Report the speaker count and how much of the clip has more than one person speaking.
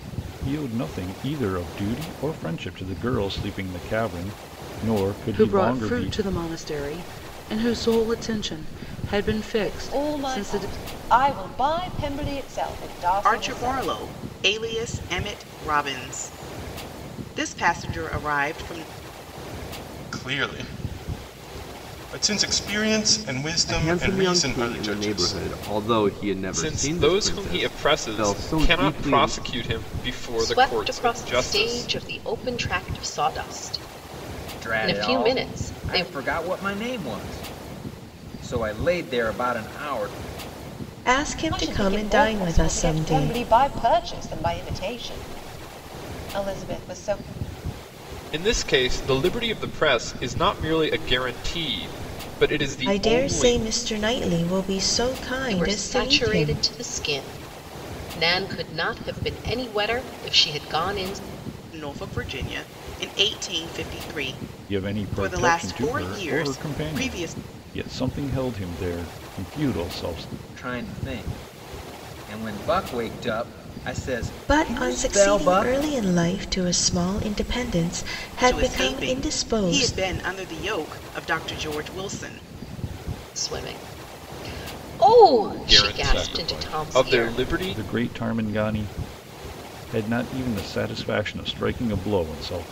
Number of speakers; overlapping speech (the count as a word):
ten, about 24%